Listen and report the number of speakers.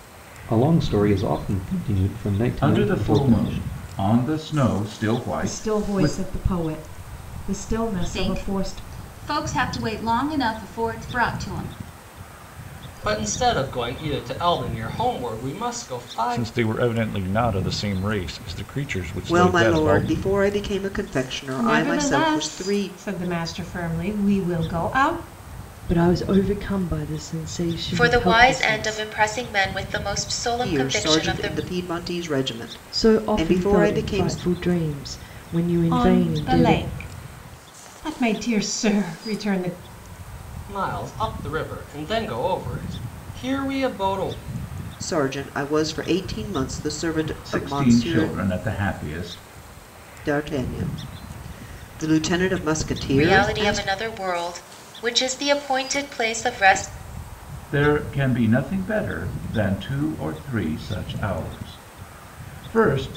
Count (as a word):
ten